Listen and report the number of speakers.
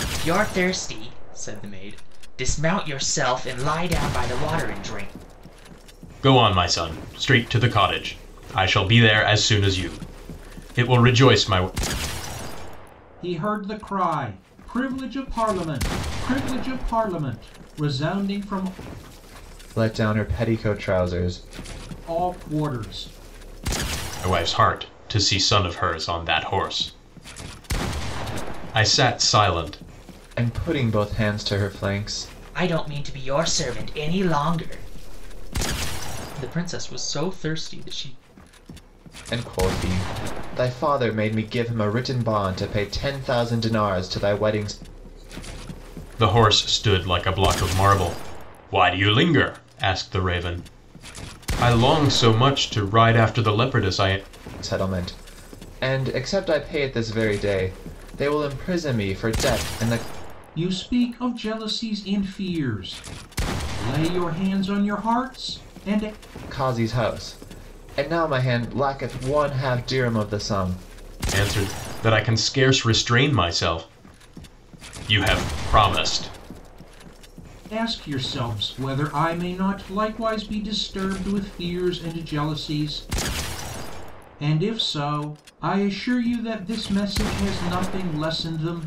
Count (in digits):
4